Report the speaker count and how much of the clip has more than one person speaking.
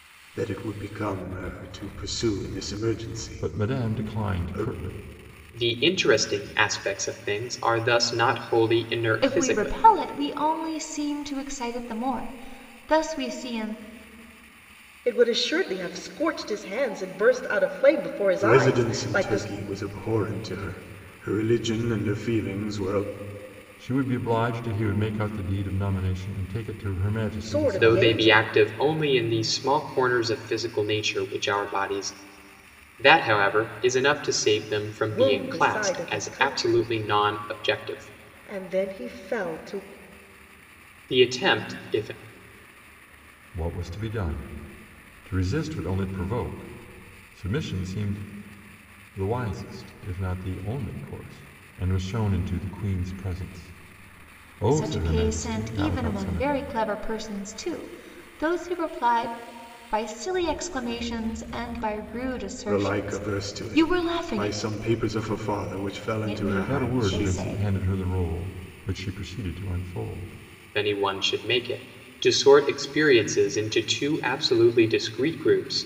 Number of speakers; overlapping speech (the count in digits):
5, about 18%